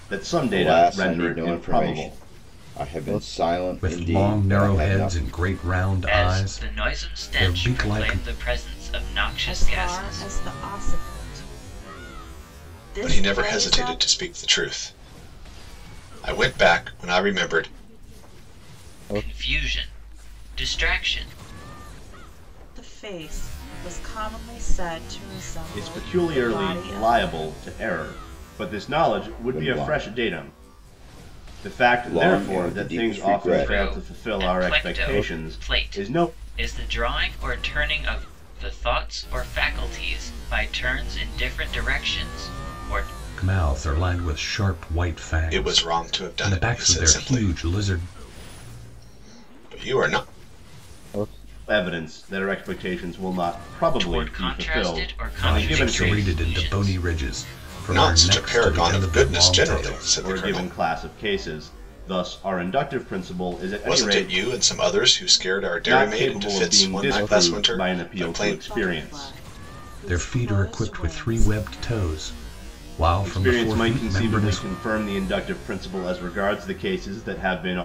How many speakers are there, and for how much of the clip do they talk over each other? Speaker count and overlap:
6, about 39%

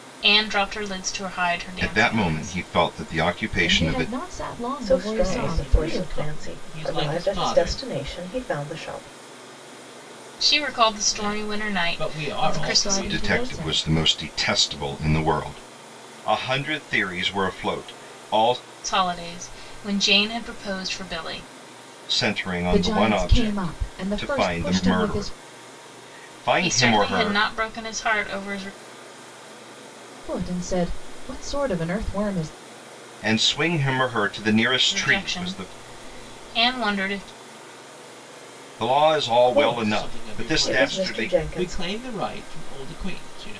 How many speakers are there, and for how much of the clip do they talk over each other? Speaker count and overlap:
5, about 32%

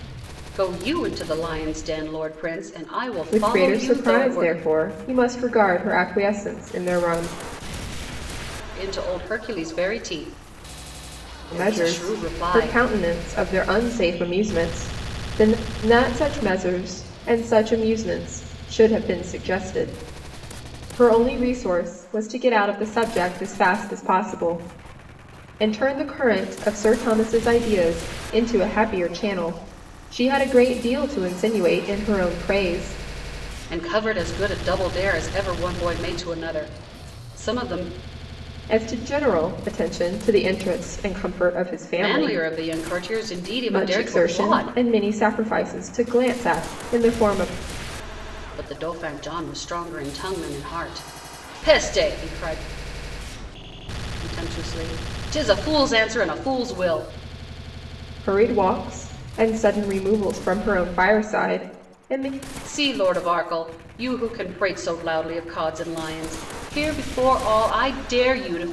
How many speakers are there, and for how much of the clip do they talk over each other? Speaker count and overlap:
2, about 6%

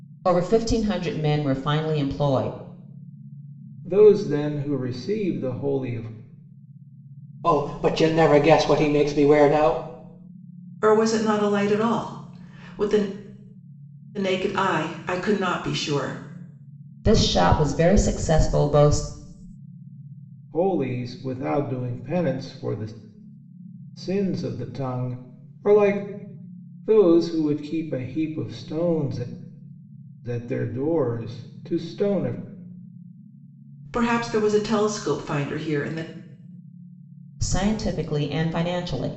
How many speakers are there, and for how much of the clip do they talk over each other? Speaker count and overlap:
4, no overlap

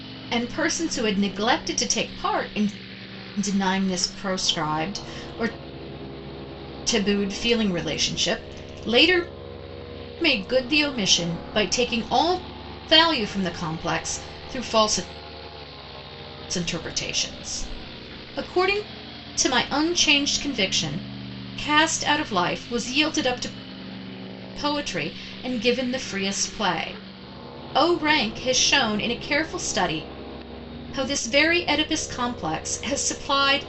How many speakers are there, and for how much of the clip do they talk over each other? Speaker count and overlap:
1, no overlap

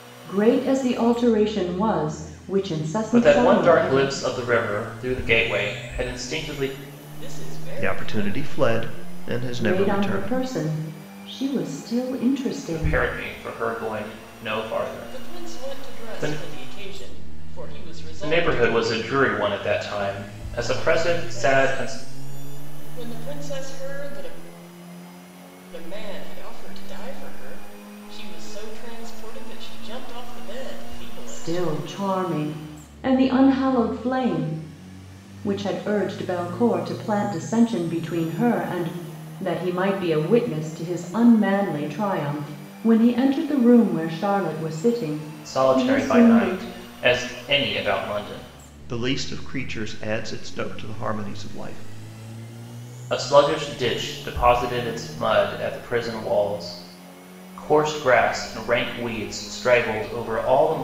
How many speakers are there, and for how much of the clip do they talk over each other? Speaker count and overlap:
4, about 13%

